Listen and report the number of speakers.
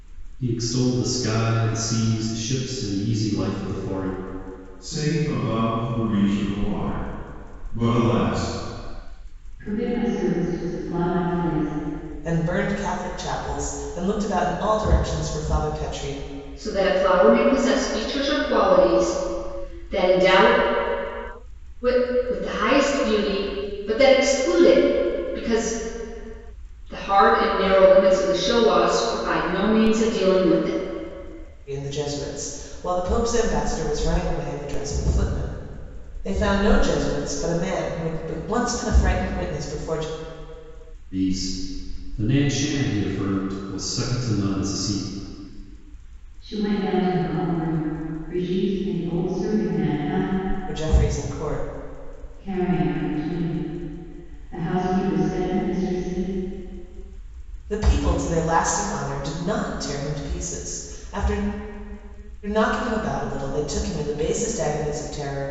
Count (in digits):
5